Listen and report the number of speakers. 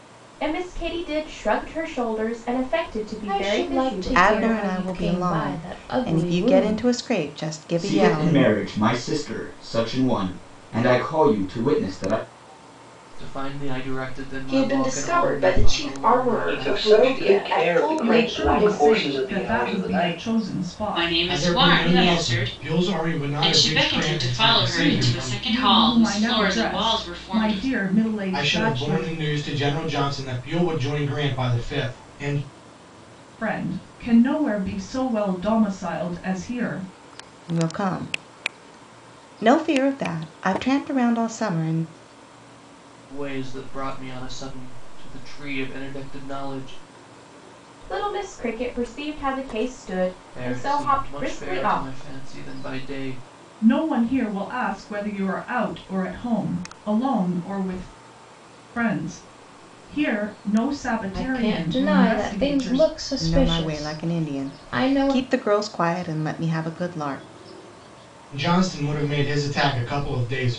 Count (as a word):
ten